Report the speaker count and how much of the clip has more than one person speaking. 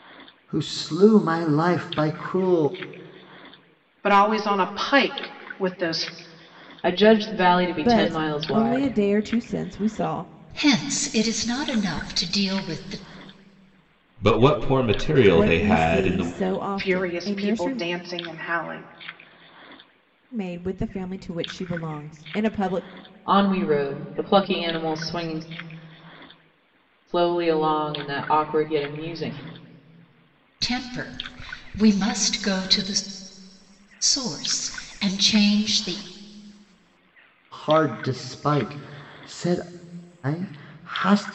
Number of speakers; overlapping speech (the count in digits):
6, about 8%